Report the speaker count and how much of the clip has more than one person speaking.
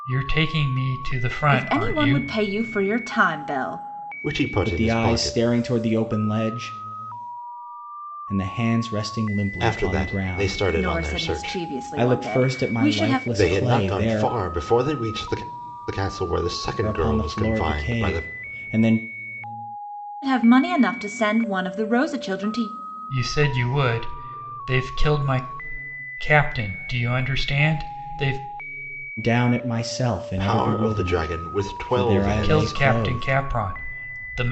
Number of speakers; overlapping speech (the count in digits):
4, about 29%